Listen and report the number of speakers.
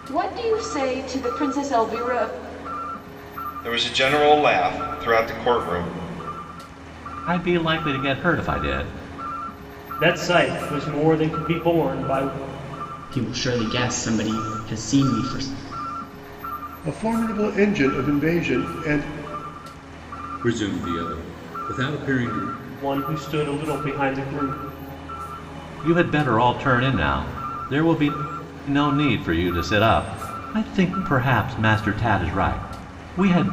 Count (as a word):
seven